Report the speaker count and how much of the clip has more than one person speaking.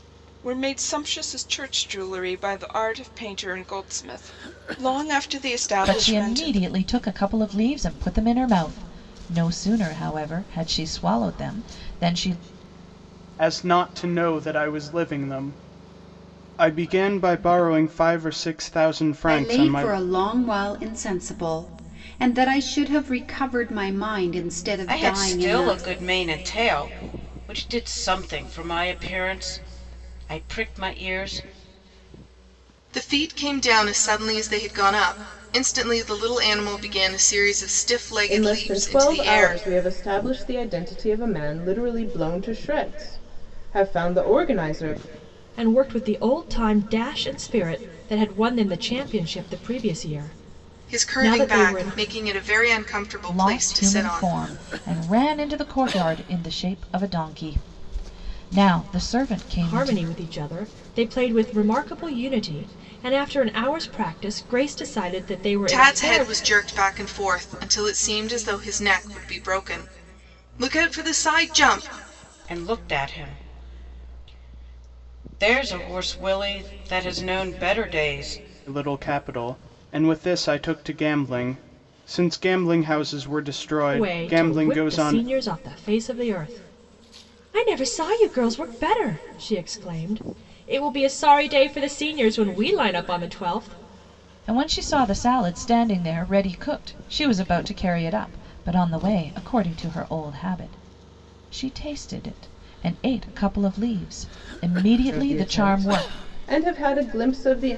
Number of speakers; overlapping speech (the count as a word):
eight, about 9%